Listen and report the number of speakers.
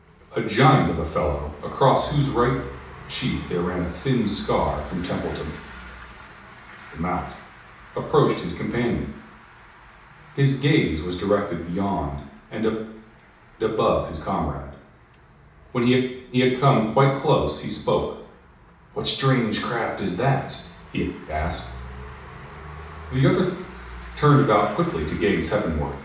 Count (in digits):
1